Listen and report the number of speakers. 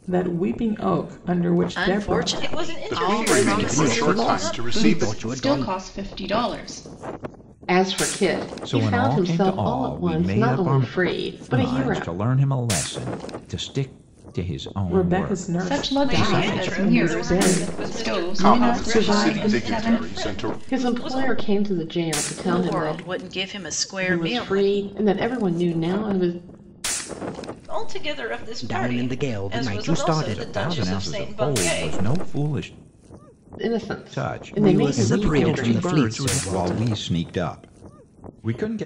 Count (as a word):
eight